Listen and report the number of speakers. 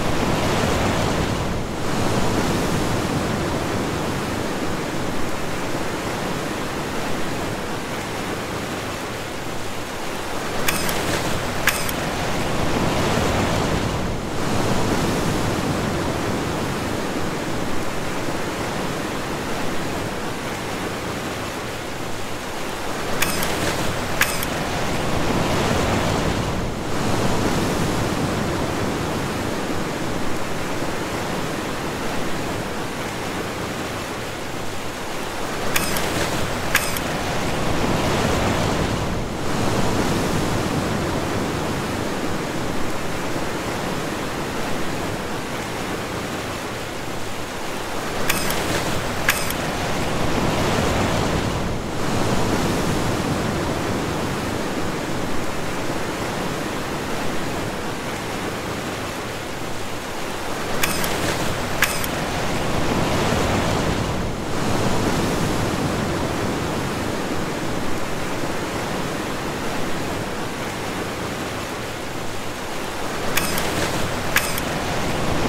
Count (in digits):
0